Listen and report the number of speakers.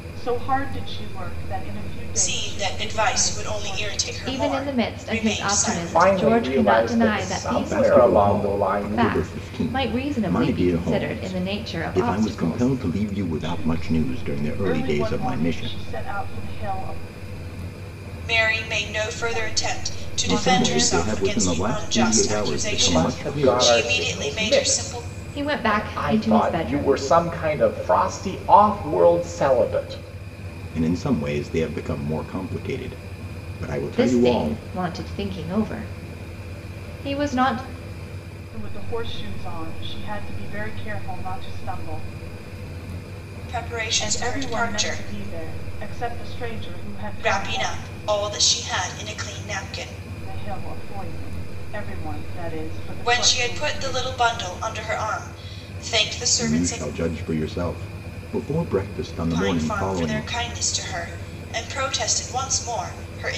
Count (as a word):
five